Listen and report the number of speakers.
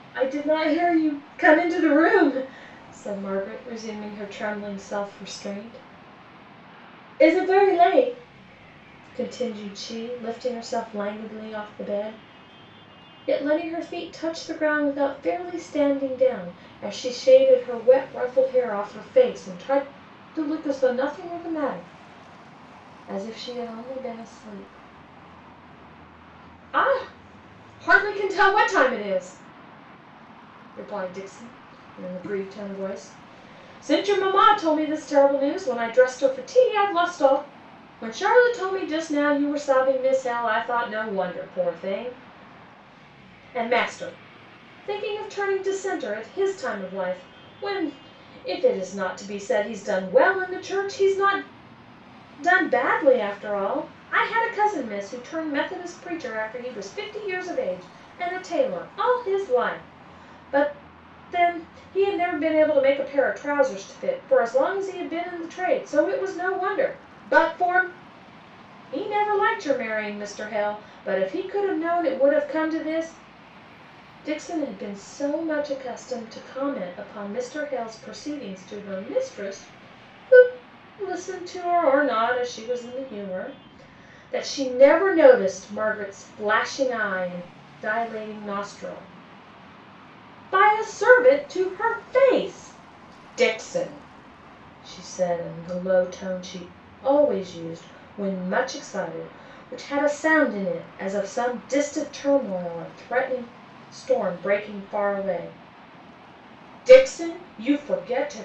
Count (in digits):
1